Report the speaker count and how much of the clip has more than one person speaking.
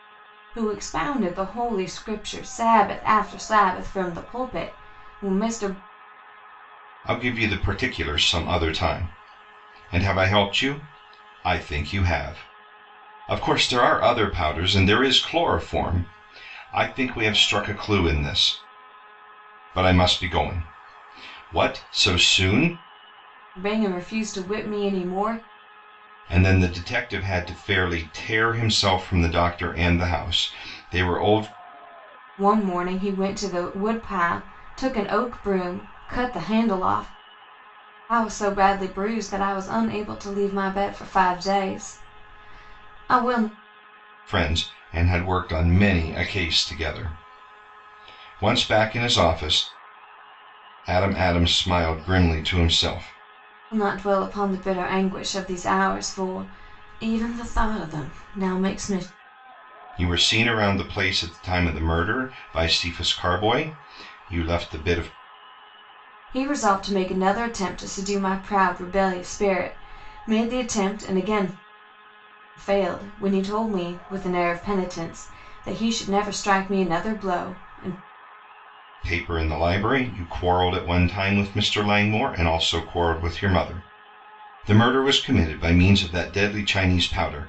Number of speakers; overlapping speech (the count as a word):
two, no overlap